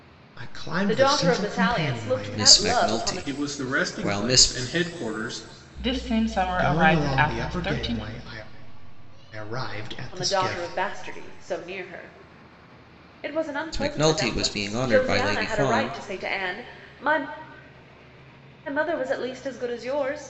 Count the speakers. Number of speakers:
5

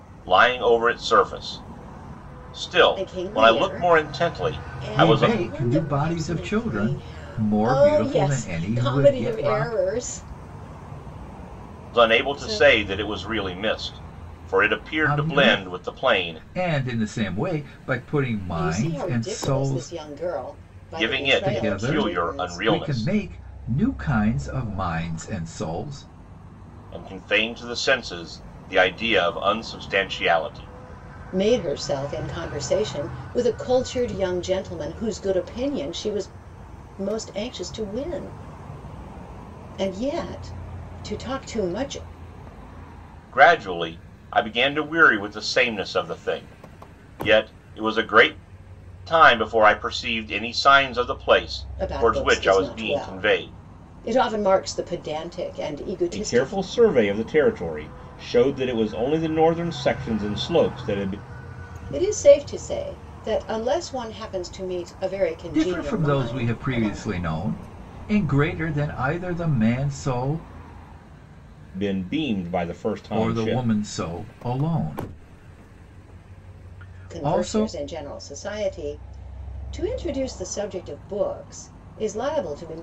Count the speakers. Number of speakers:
3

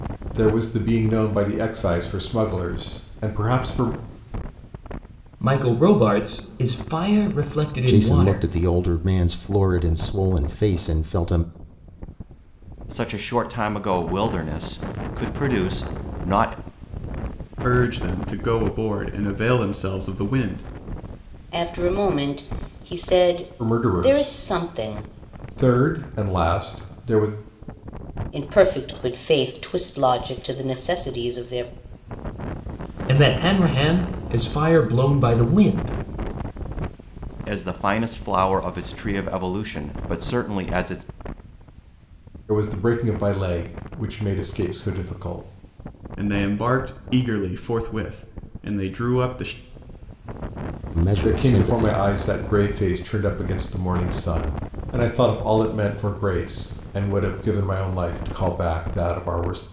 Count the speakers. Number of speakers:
6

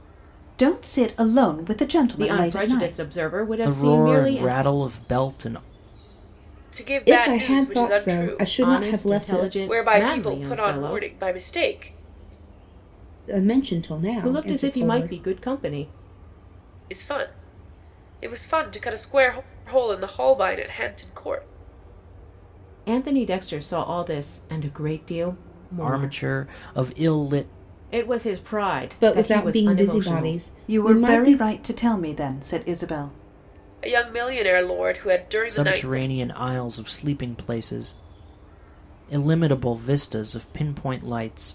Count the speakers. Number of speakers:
5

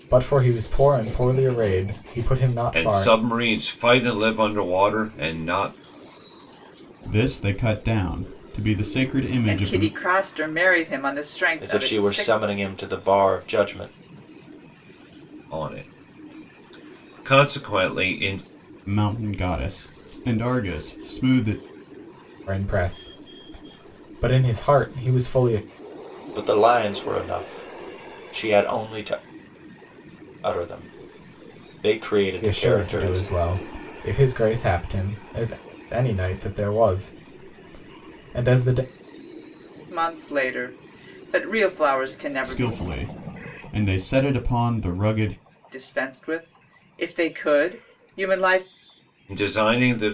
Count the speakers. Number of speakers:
5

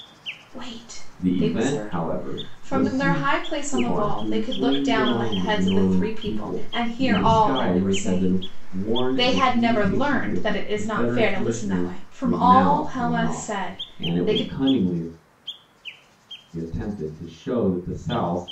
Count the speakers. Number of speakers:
2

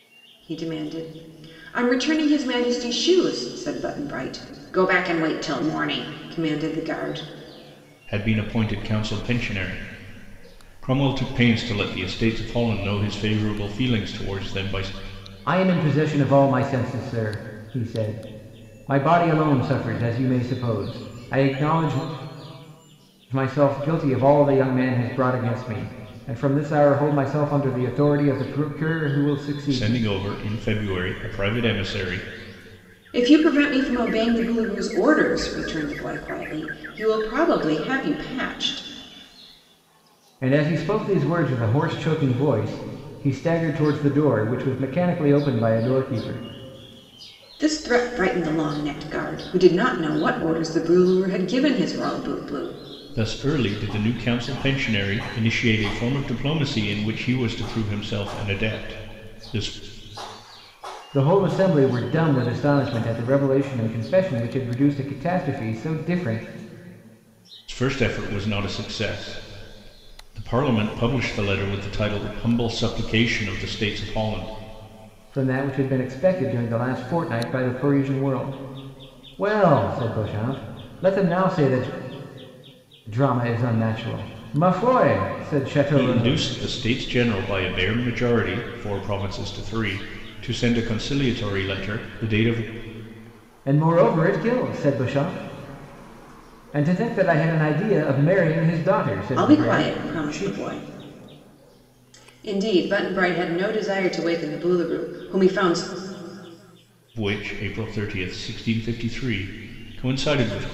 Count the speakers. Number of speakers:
3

